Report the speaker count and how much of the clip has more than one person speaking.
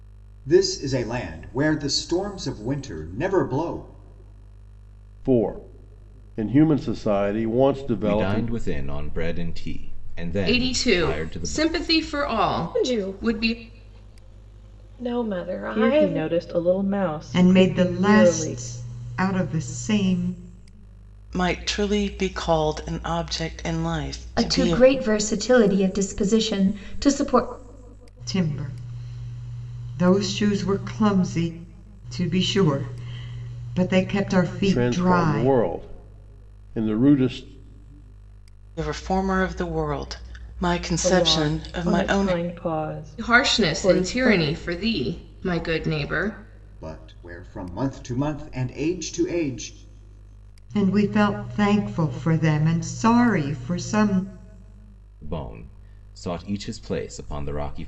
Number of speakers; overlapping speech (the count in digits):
9, about 15%